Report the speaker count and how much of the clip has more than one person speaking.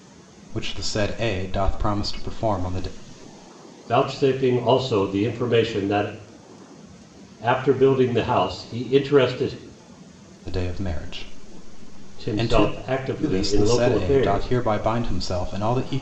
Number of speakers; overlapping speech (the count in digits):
2, about 12%